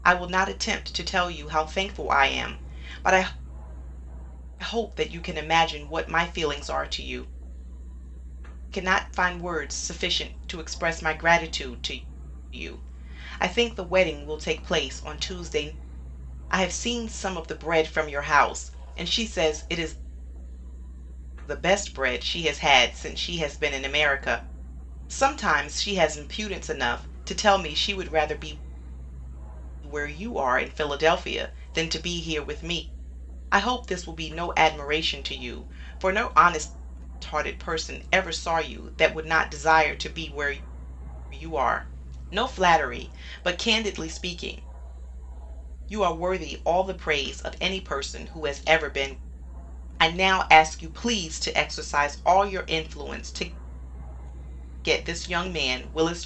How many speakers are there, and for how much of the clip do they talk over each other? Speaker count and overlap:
1, no overlap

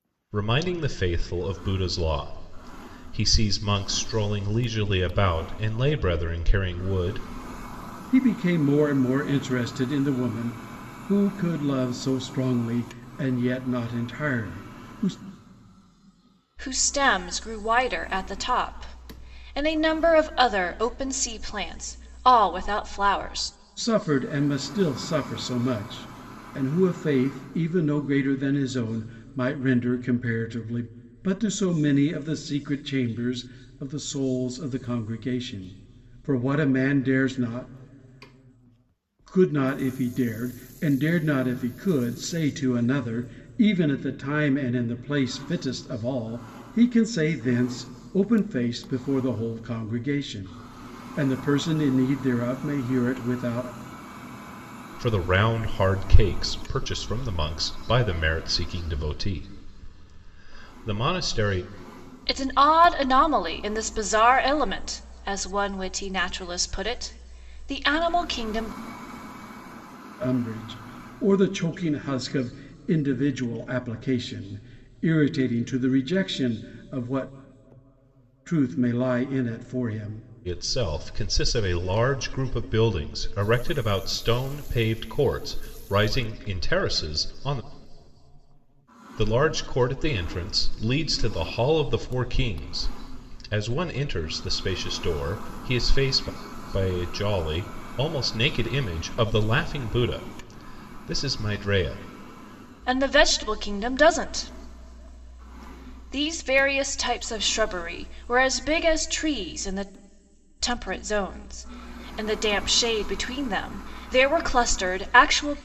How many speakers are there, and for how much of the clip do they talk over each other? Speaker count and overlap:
3, no overlap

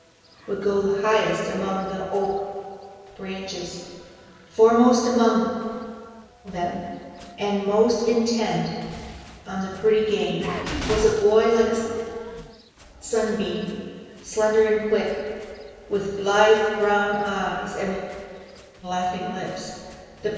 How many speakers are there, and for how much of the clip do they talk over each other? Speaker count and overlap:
1, no overlap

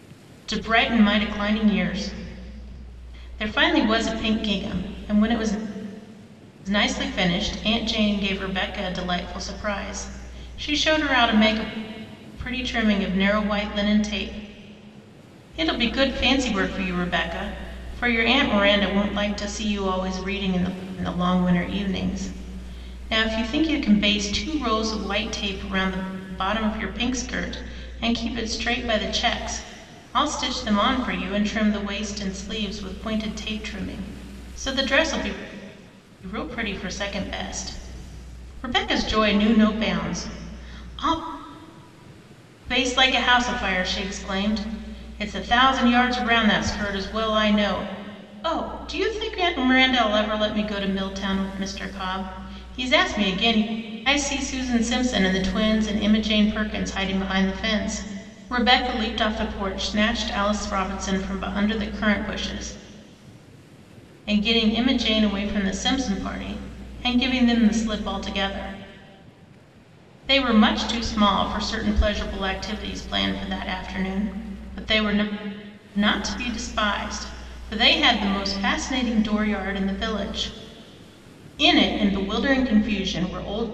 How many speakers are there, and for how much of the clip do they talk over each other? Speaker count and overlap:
1, no overlap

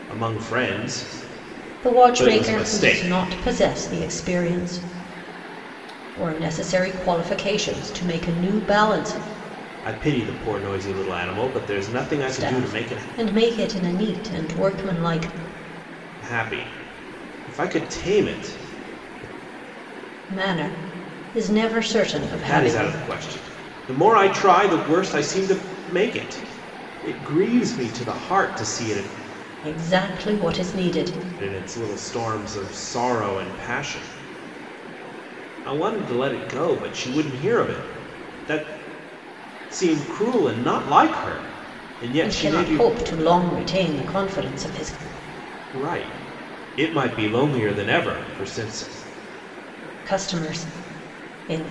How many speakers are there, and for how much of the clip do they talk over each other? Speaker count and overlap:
2, about 7%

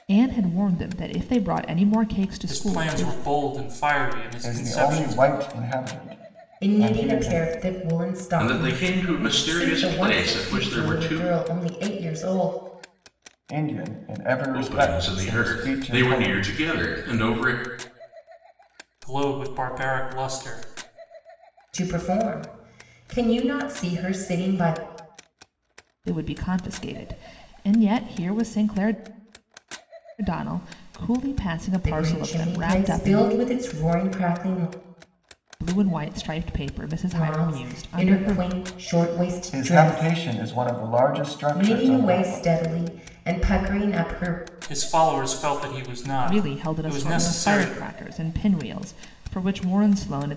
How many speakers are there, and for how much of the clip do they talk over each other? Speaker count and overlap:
5, about 27%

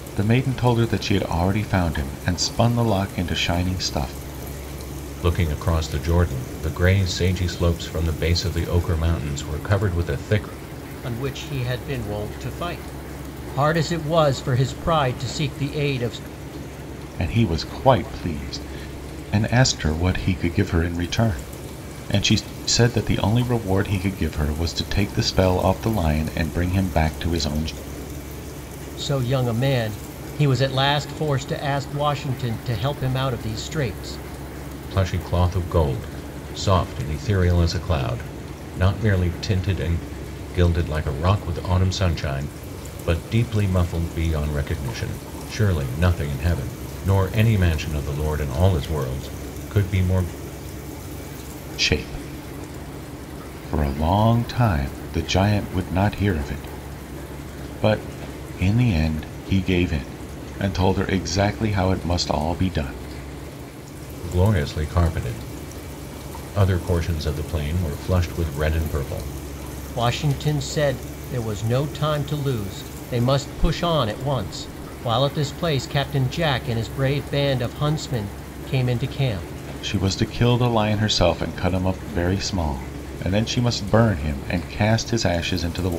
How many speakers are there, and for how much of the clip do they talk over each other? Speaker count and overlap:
3, no overlap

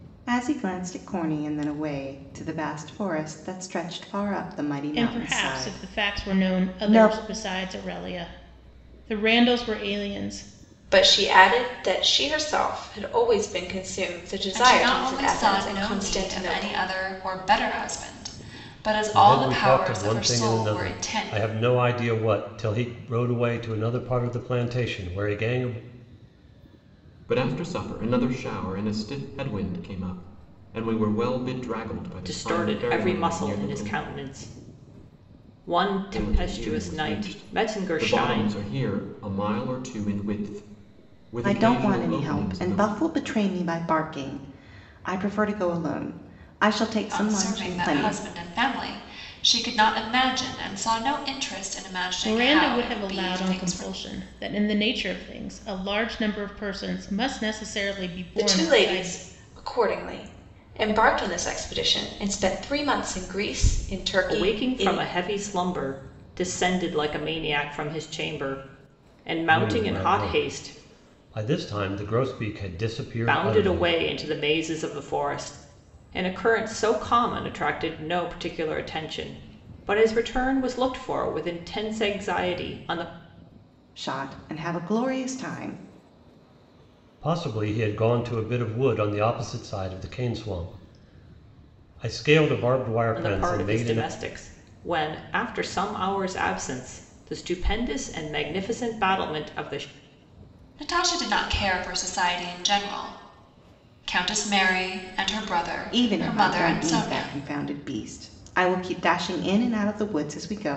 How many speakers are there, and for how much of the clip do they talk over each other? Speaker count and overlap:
7, about 19%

